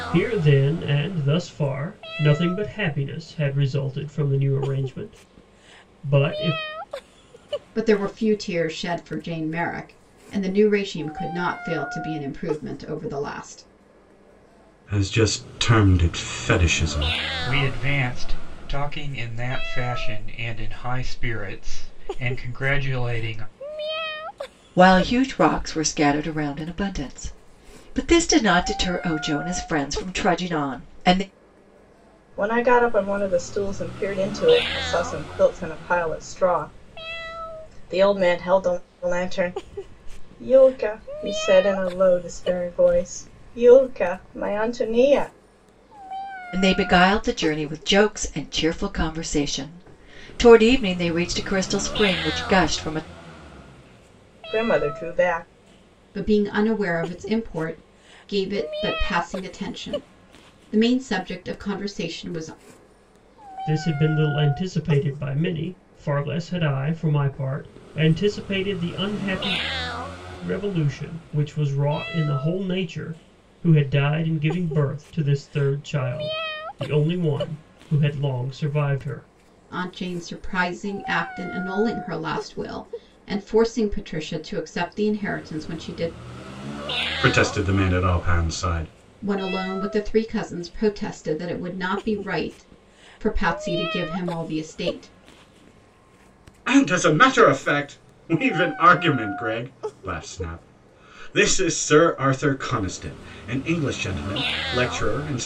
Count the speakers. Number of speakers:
six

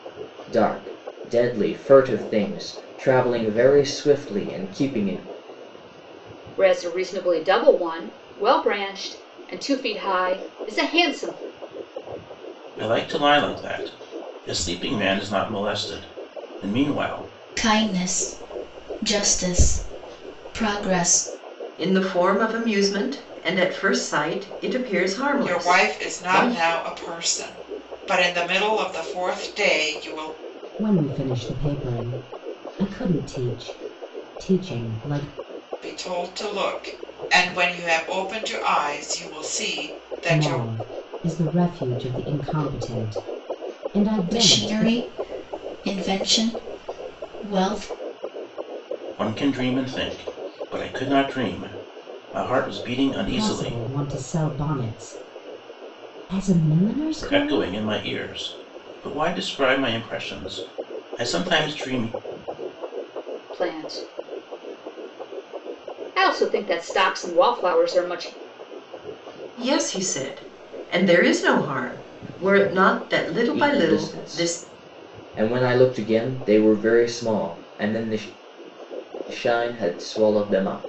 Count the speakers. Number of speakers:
seven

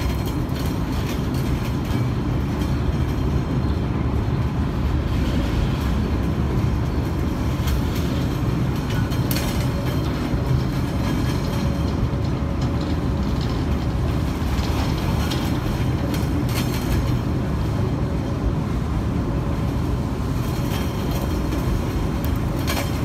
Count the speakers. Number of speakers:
zero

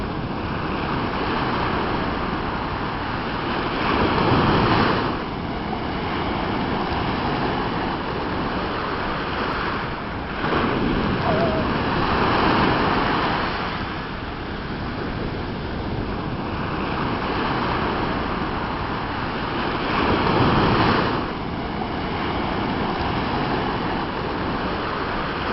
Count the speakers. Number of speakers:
zero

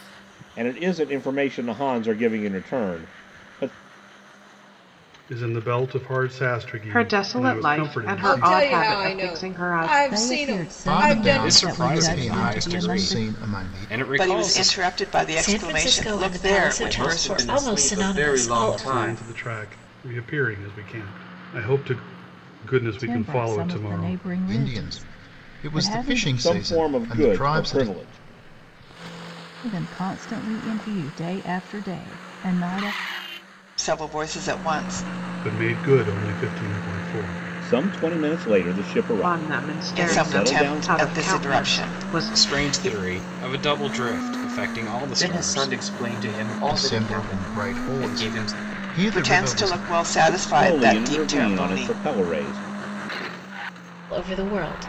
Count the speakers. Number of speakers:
ten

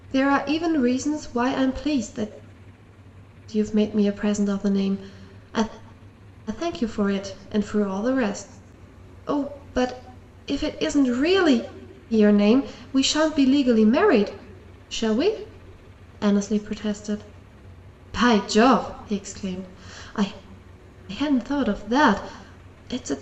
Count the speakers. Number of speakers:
one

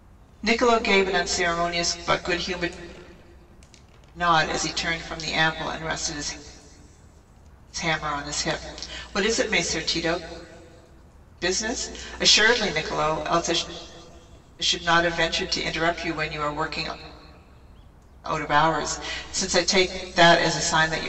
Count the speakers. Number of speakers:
one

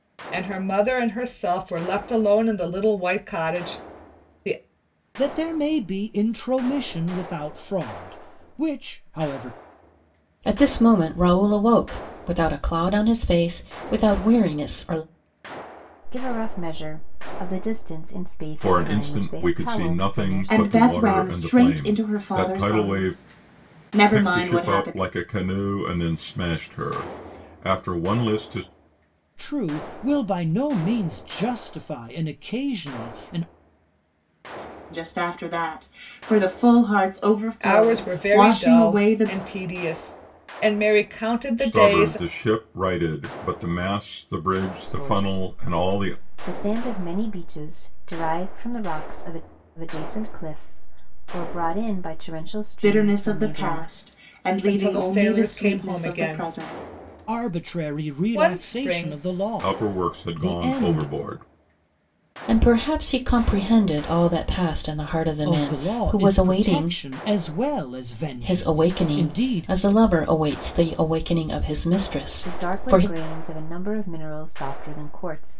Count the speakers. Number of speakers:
six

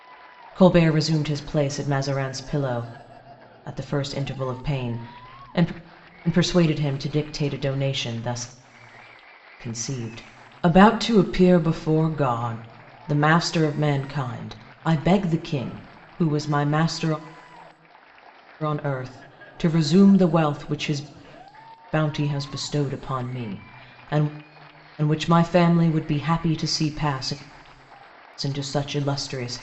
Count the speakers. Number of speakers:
one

